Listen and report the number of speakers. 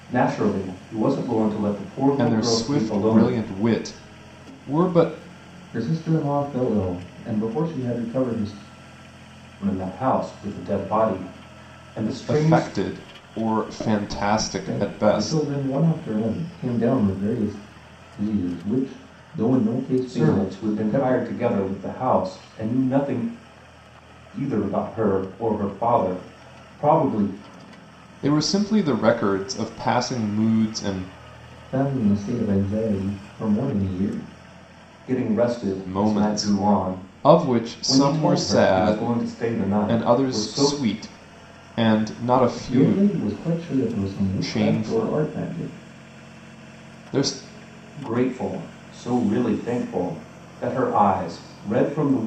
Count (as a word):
three